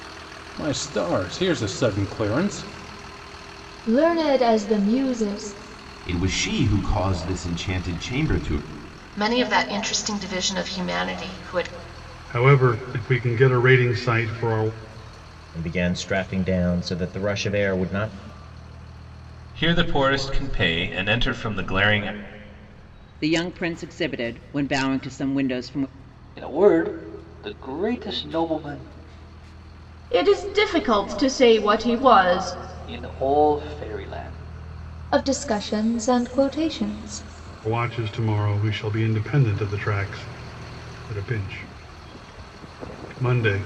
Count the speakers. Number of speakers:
10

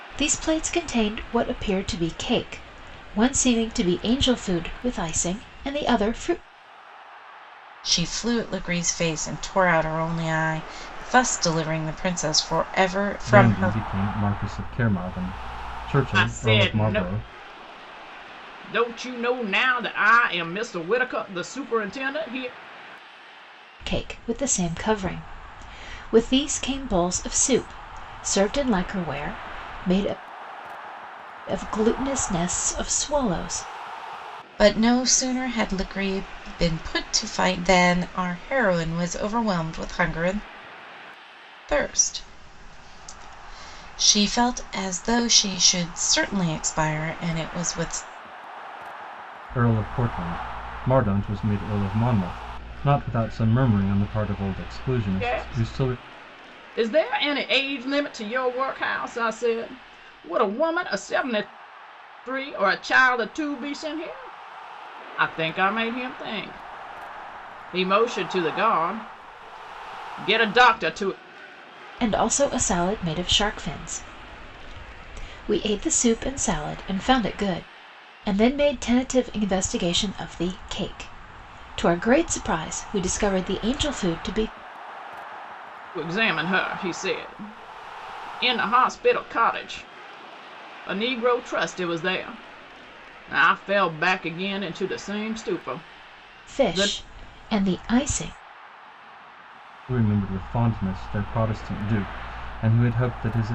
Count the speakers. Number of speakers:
4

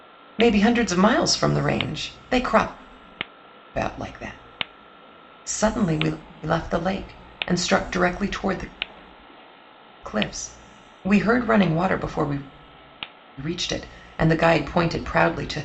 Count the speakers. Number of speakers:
1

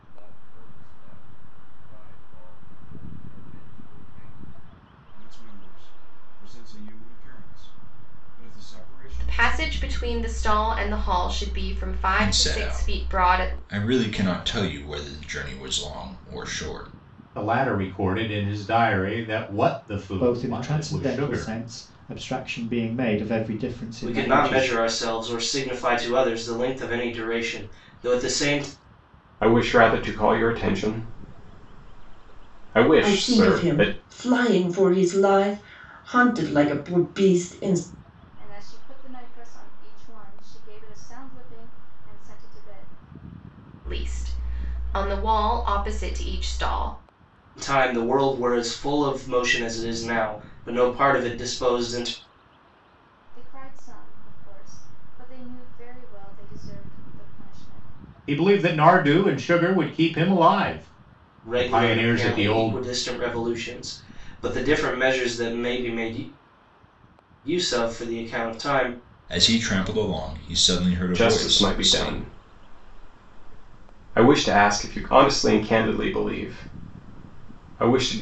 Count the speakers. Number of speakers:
10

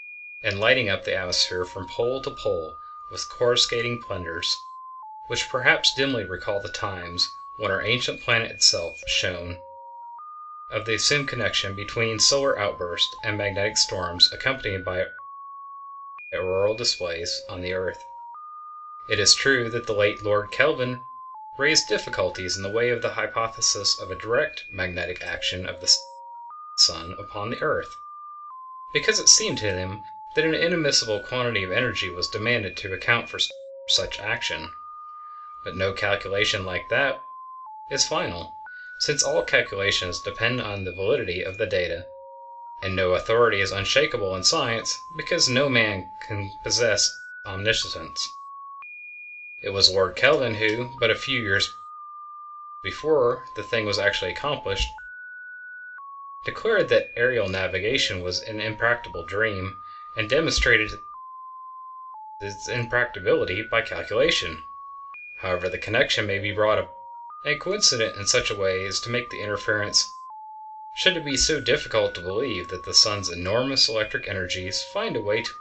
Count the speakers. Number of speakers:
1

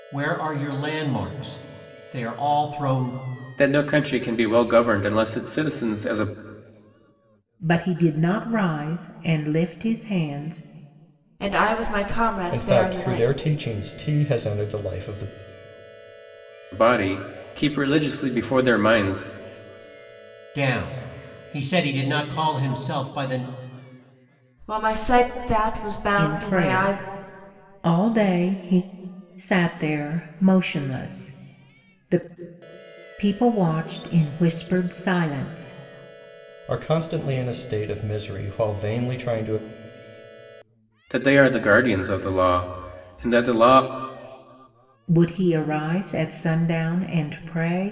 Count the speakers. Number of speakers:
5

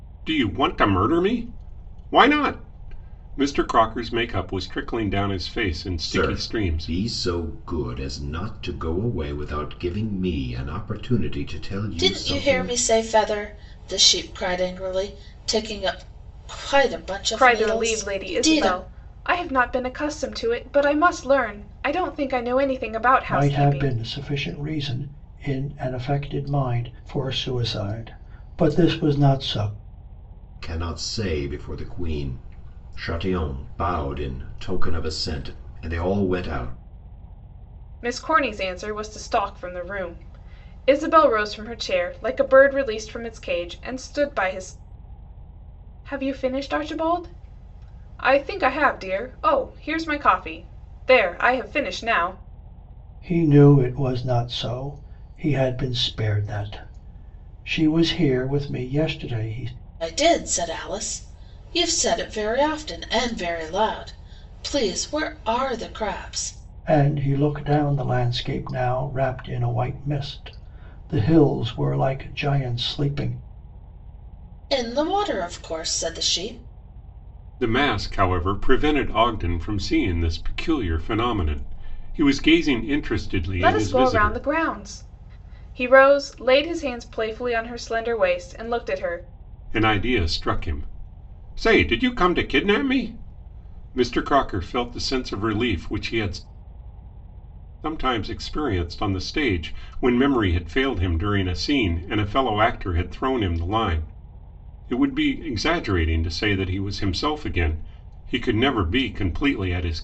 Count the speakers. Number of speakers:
5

